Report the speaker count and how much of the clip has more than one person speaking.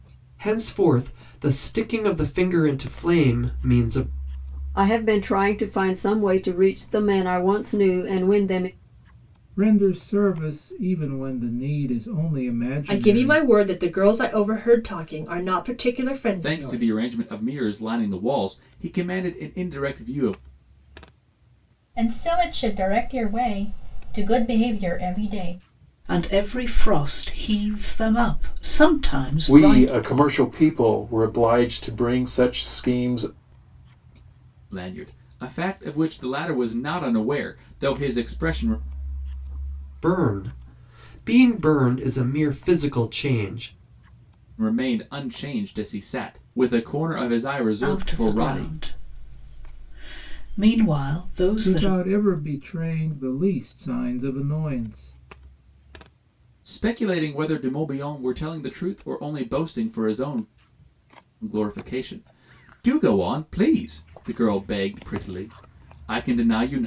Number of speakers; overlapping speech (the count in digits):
8, about 4%